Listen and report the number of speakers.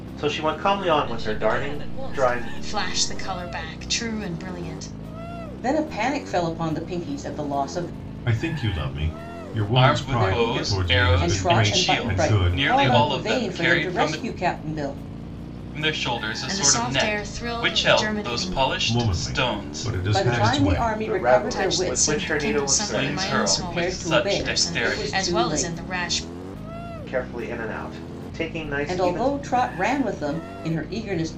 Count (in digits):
6